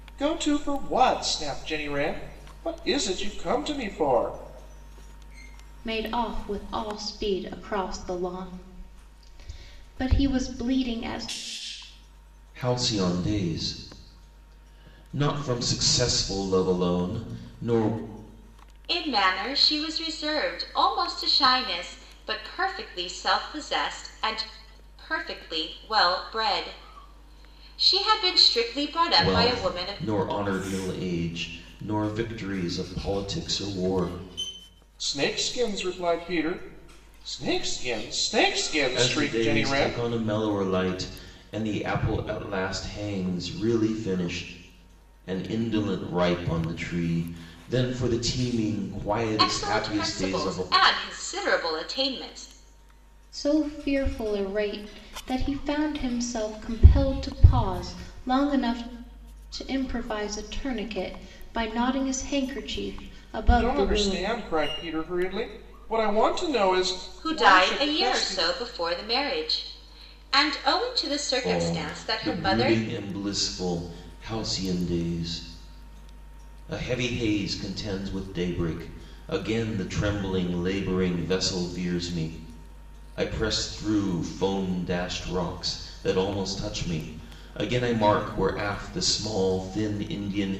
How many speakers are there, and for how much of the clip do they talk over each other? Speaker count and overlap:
4, about 8%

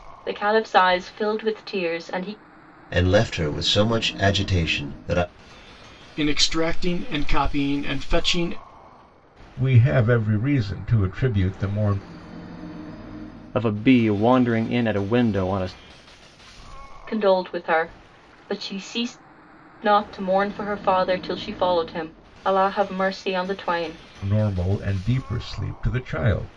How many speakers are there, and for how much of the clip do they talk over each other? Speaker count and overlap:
5, no overlap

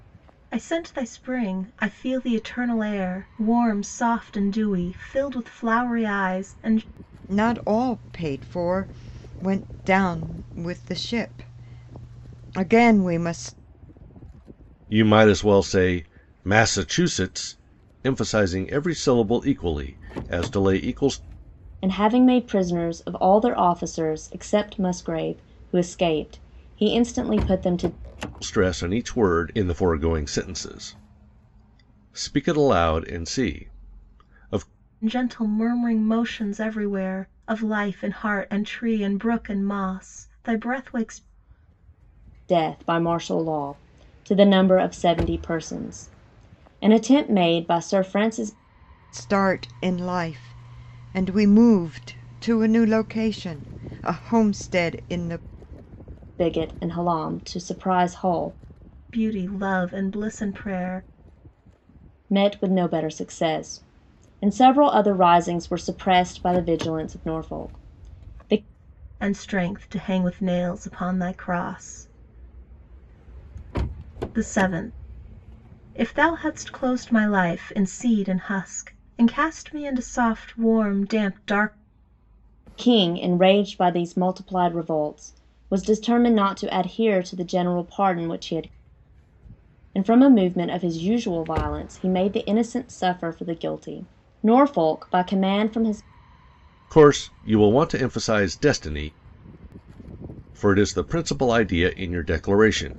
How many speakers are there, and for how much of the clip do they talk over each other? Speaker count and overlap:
4, no overlap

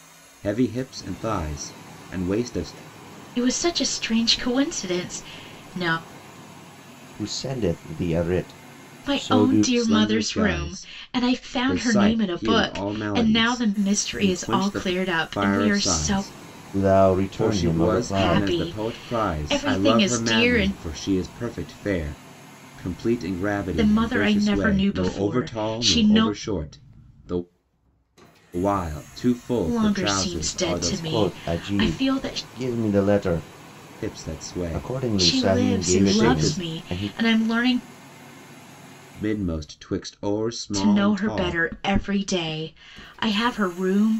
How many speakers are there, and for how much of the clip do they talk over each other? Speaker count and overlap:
3, about 45%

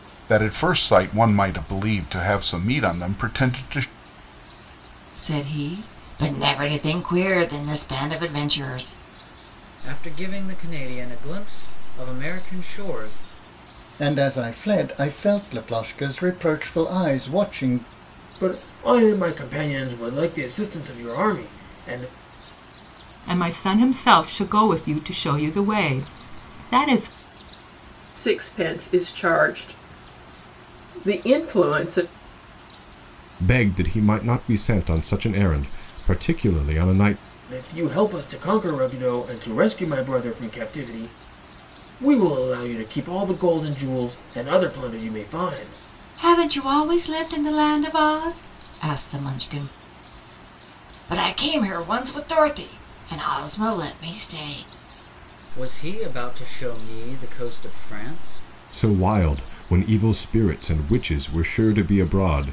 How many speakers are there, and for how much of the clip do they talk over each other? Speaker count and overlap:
8, no overlap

